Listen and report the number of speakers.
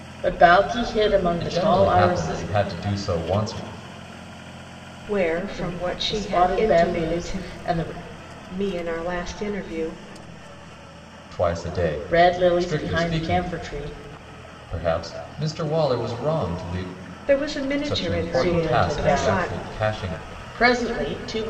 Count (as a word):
three